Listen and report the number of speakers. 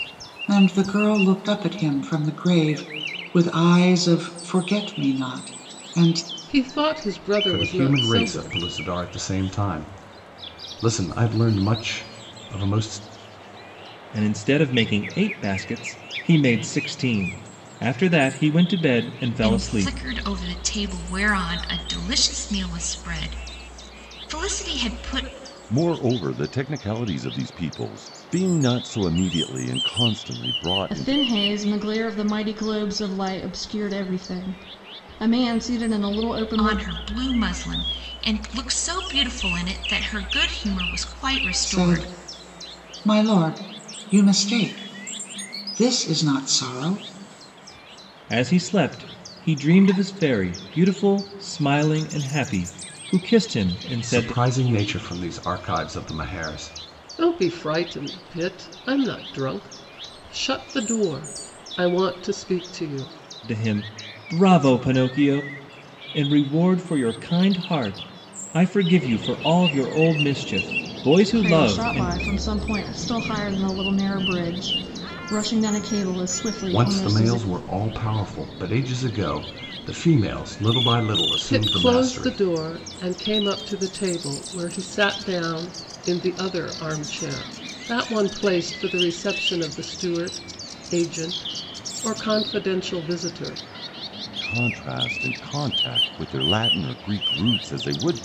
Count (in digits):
7